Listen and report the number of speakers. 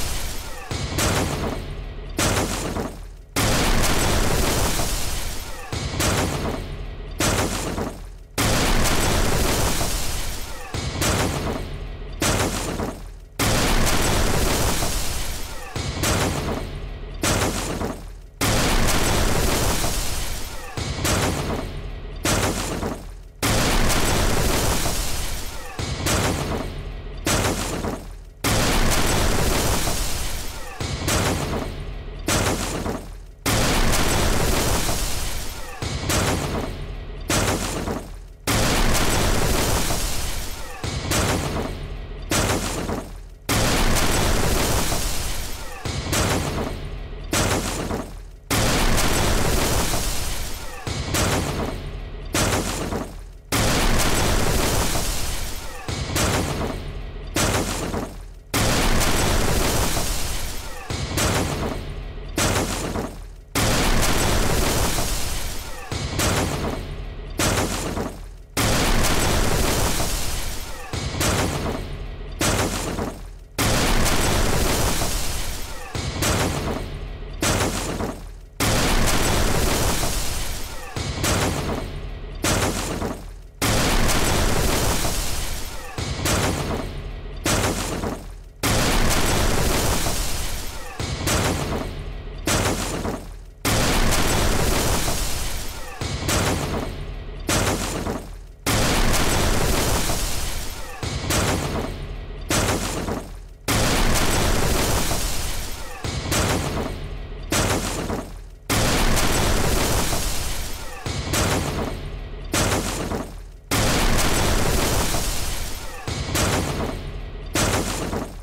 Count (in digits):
0